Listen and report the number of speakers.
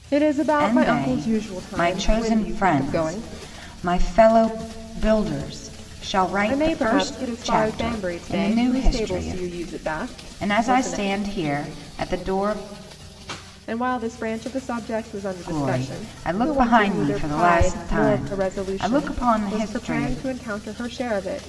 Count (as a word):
two